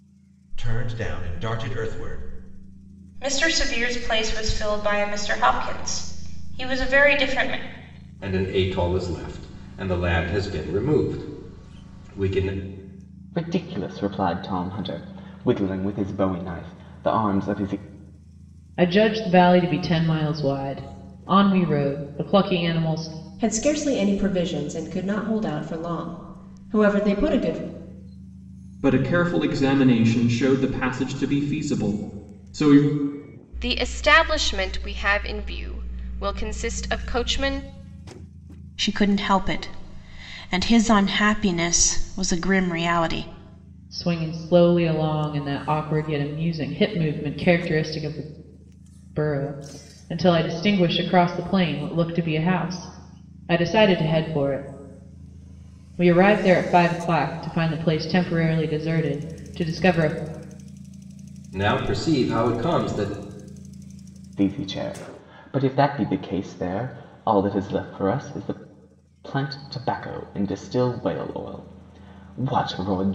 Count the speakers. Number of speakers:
nine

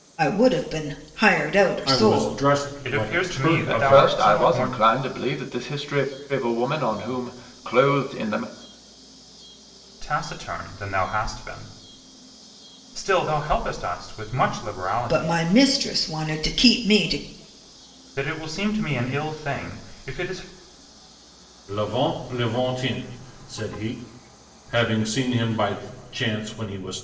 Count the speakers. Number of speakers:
four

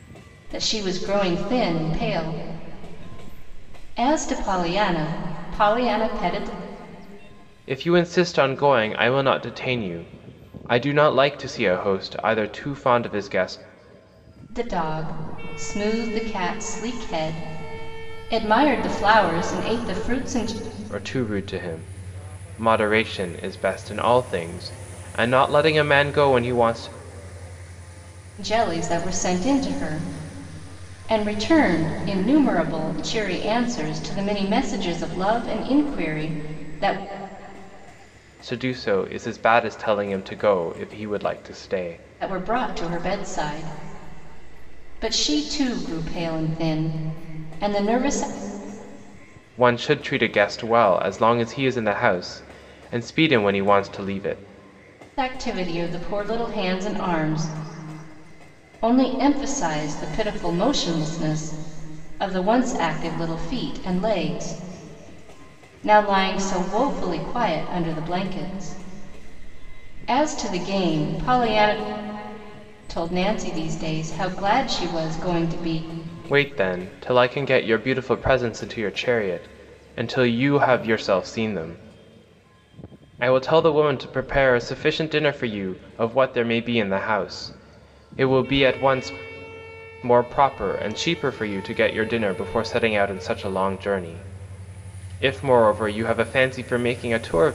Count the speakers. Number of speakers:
two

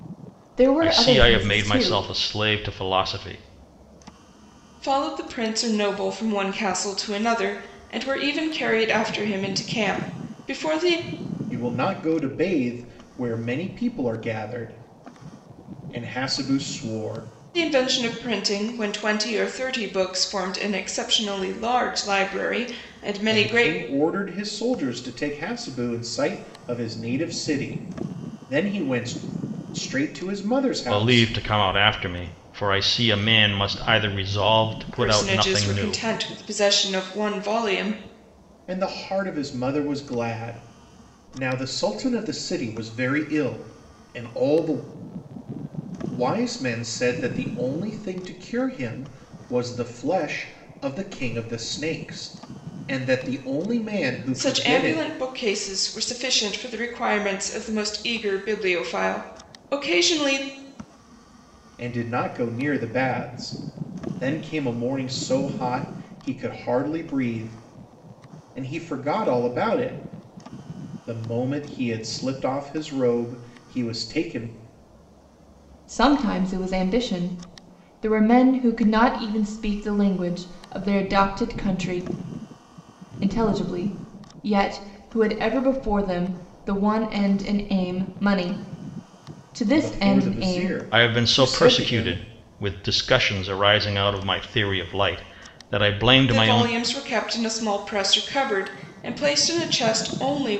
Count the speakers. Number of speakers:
four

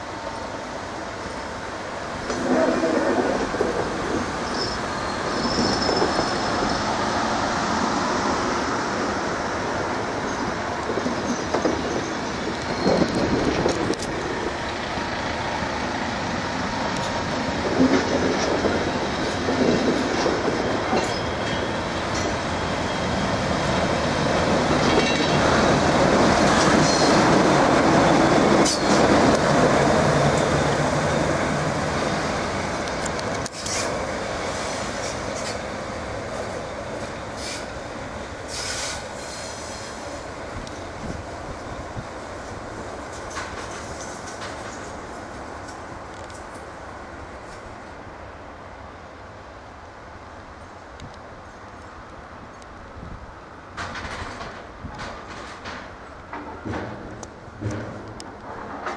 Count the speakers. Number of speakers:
zero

